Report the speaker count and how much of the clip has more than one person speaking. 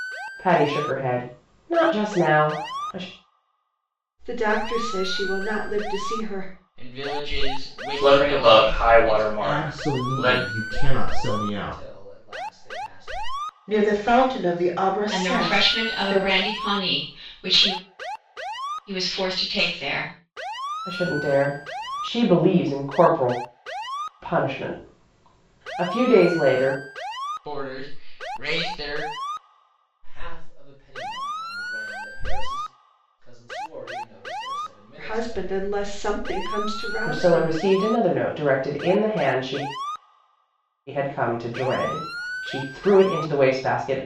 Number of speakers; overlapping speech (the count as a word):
eight, about 14%